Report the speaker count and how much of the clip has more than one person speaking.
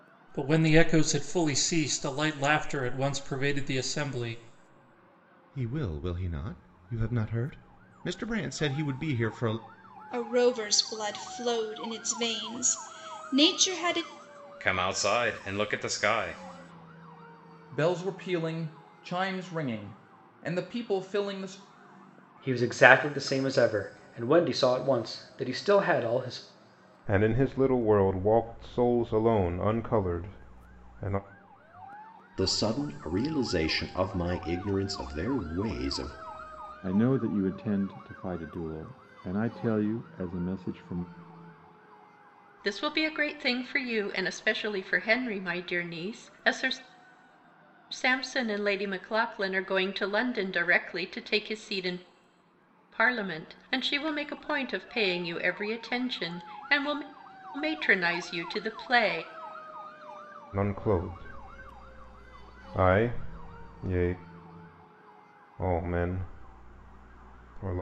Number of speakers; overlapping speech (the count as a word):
ten, no overlap